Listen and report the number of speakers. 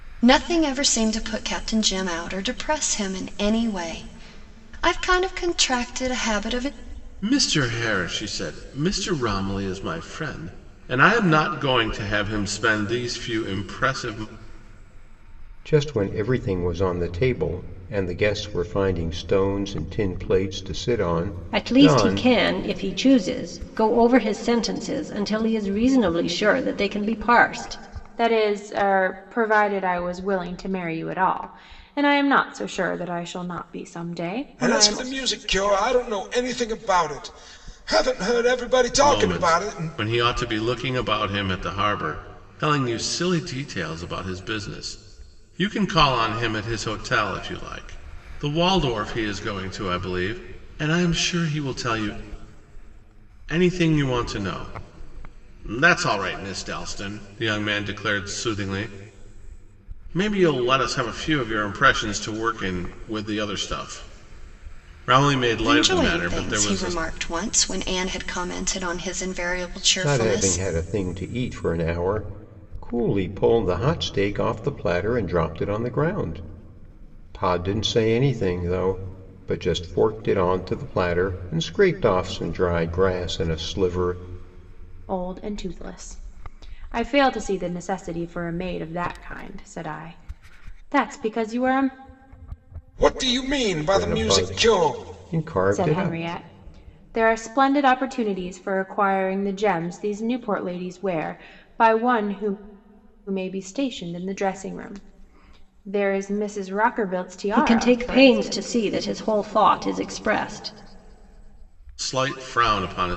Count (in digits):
6